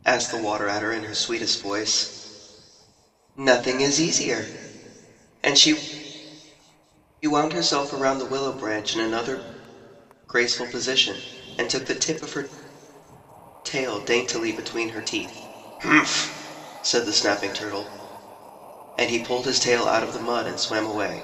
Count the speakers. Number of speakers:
1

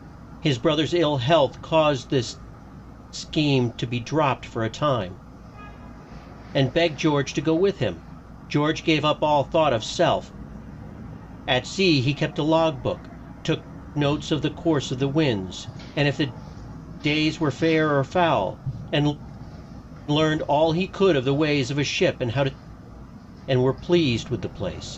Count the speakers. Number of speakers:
1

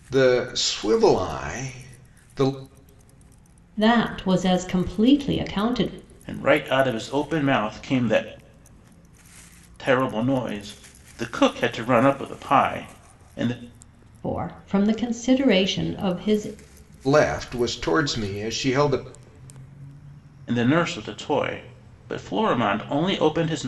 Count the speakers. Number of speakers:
3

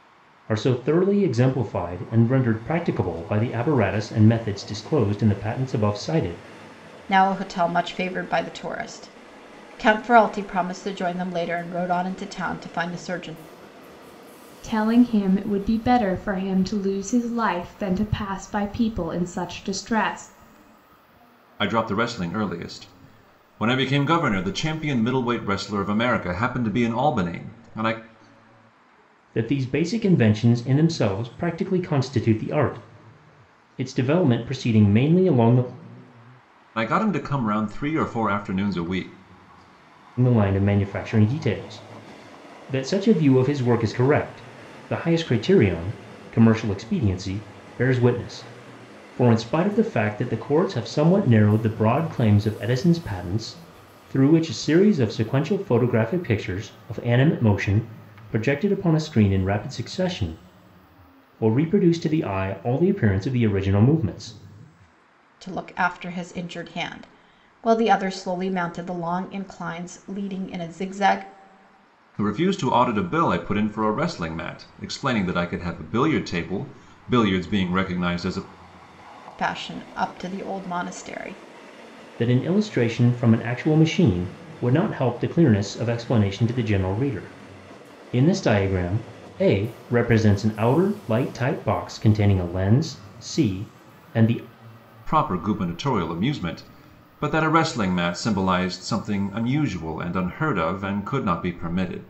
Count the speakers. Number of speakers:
4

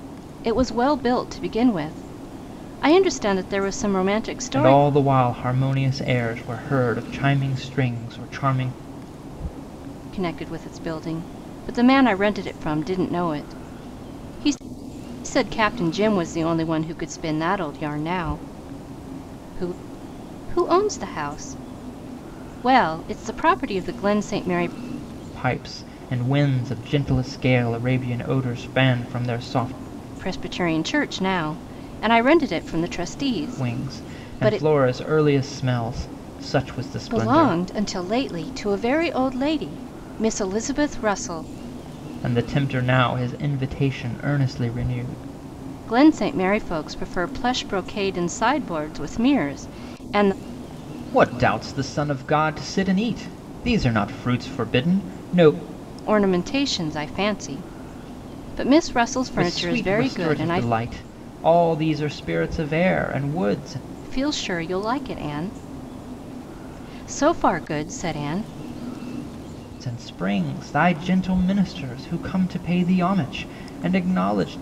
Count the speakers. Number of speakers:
2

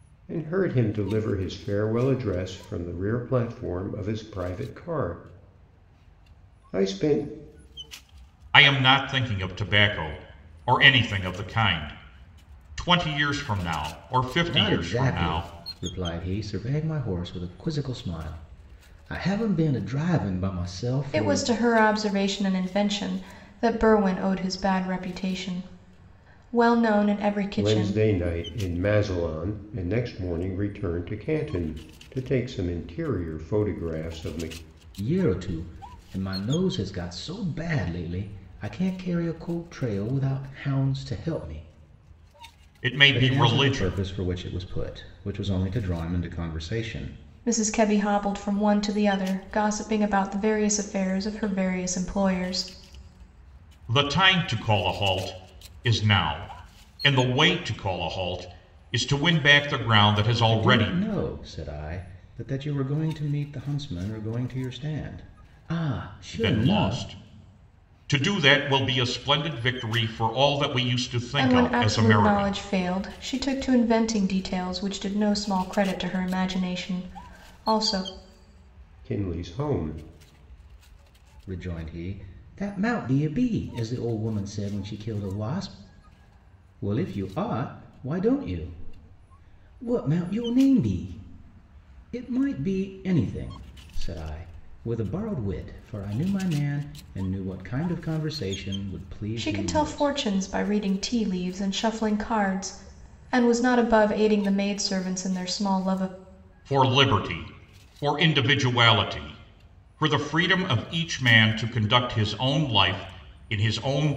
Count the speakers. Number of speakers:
4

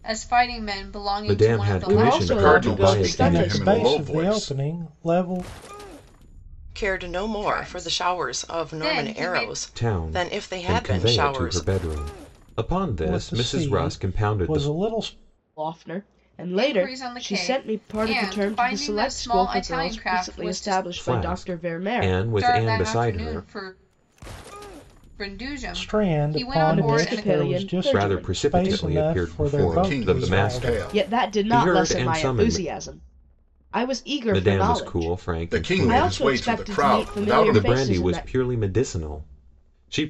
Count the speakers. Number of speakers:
6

